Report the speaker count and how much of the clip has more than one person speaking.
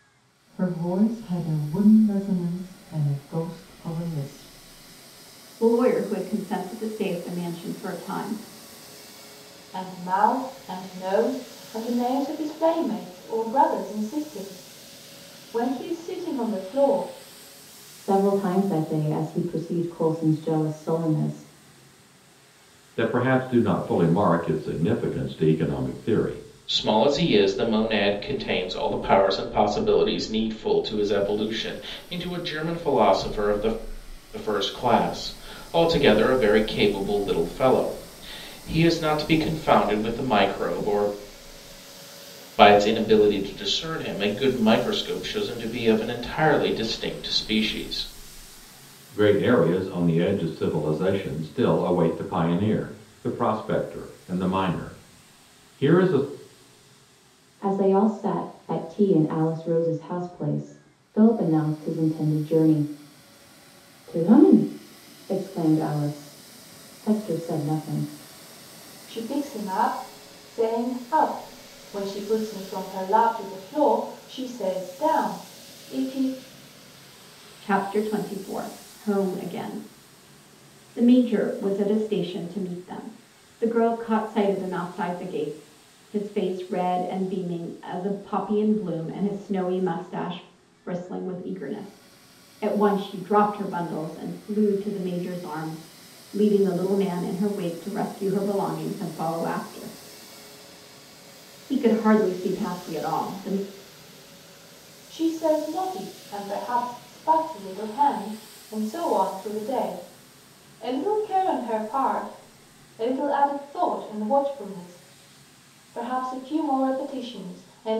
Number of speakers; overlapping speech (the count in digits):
6, no overlap